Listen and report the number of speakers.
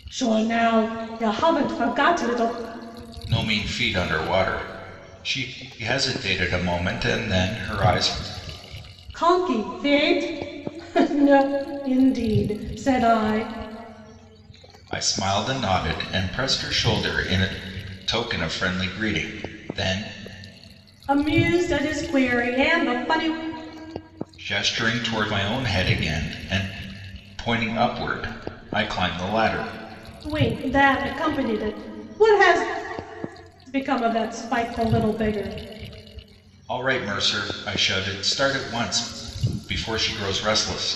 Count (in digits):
2